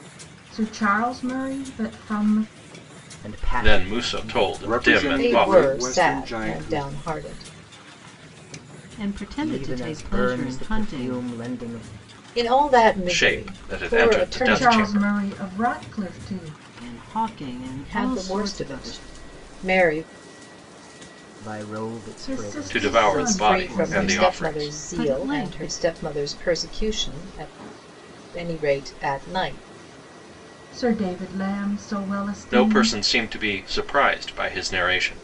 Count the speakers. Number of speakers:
6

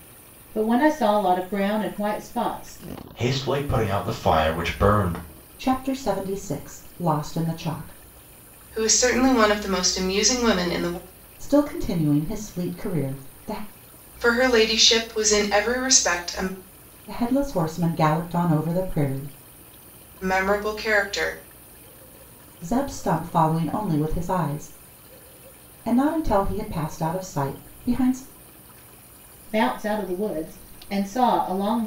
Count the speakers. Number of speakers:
4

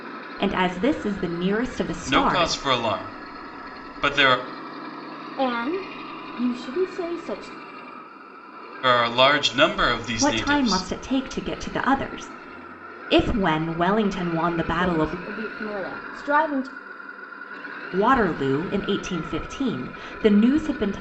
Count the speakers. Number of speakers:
3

